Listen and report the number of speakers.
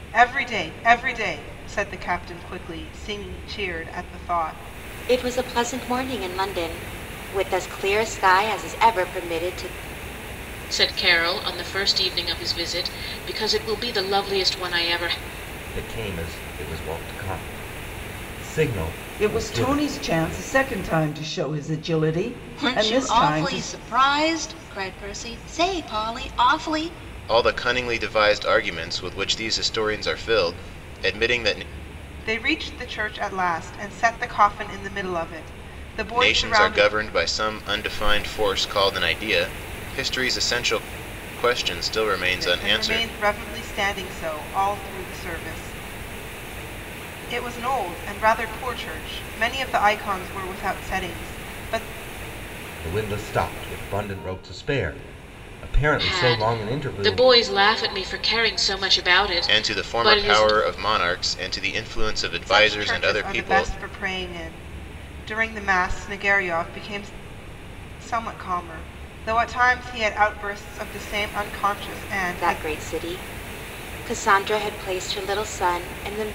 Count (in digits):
7